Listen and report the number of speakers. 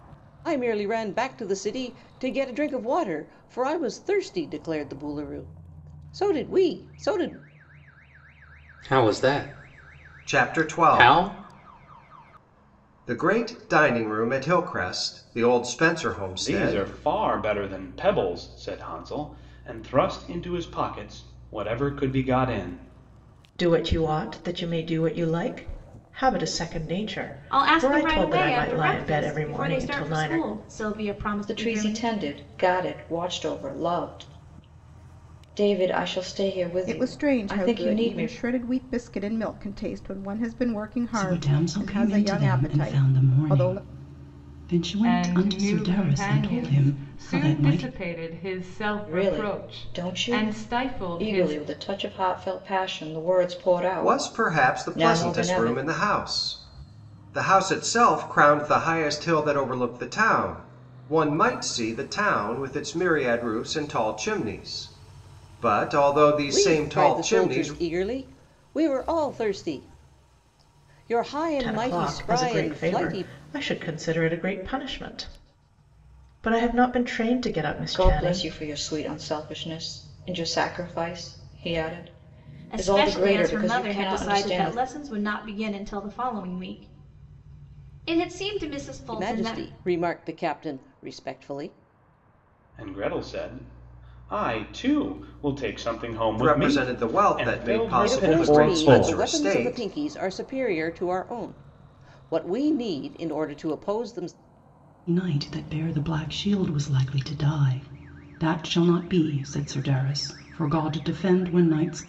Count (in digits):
10